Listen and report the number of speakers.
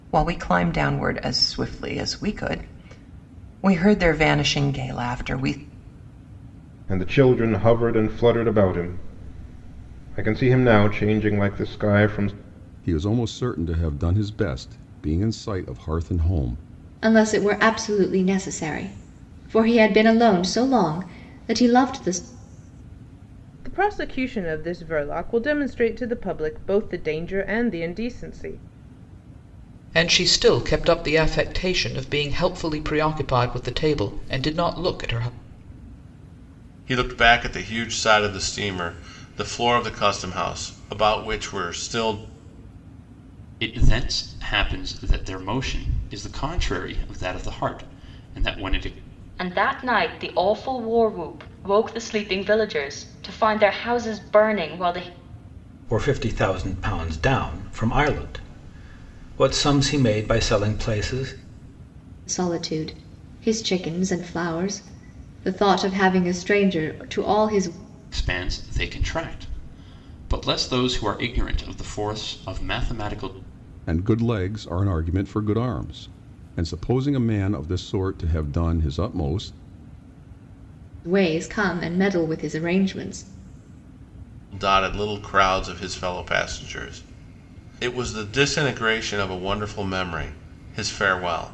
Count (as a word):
ten